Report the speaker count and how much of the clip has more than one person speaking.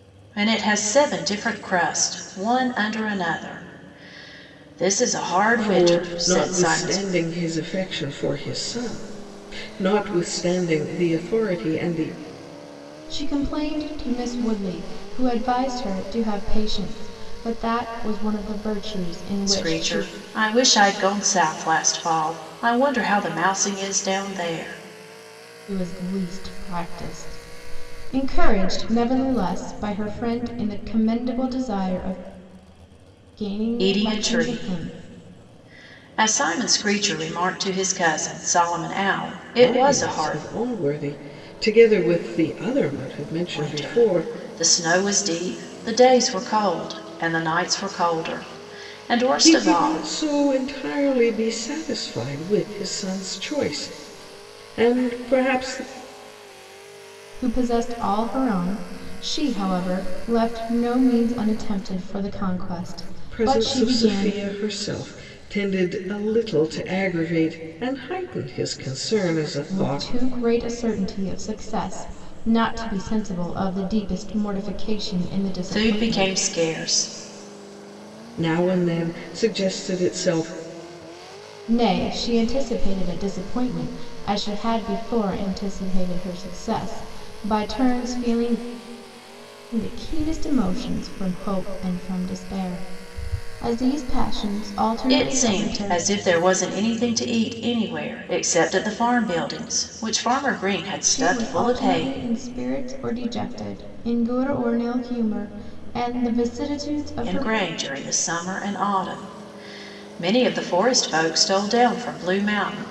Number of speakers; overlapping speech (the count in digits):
3, about 9%